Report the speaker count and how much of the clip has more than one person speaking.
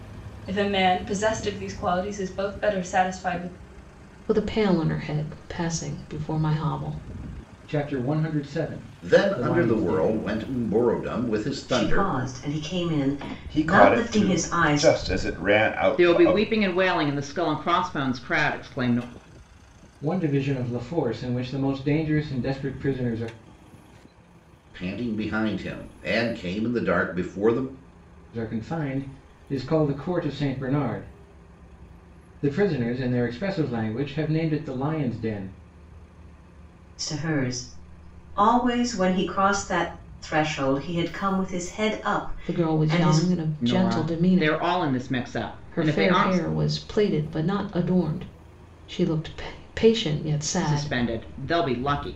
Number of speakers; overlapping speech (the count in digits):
7, about 13%